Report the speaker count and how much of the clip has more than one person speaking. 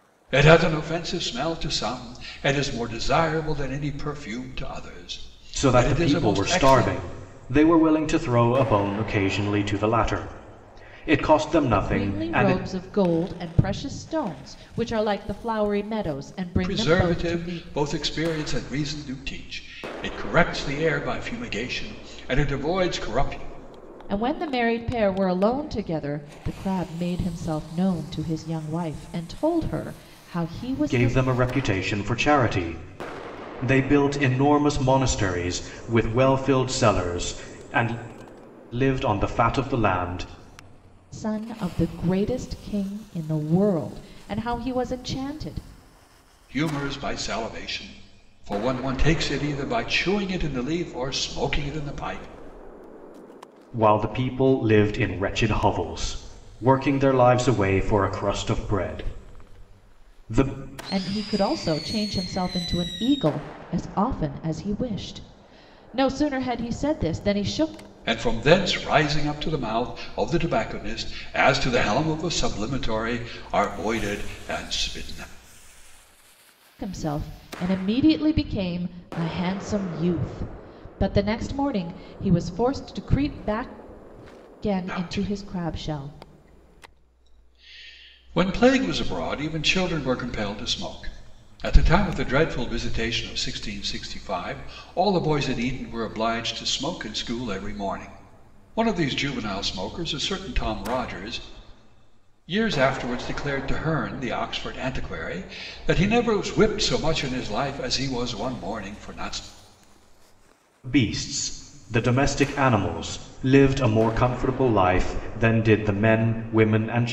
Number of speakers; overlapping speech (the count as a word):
three, about 4%